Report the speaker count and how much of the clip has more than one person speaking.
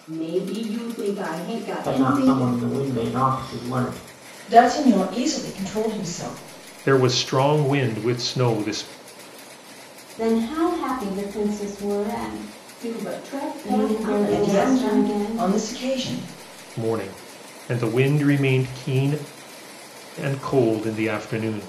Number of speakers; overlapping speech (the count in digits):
5, about 12%